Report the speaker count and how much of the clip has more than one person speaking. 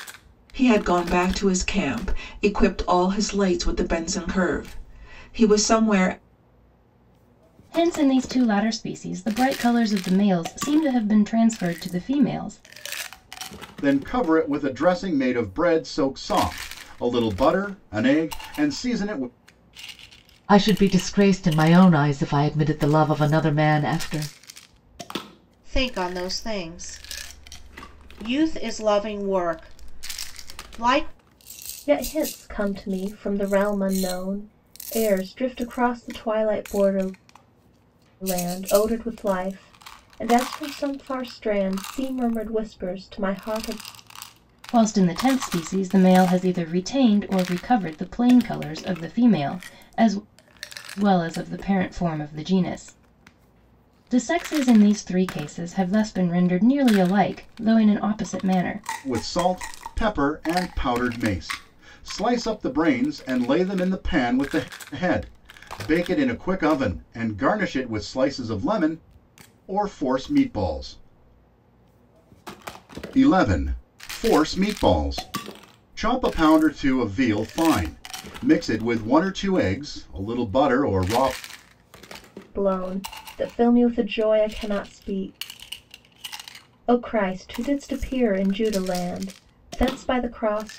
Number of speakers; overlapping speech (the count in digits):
6, no overlap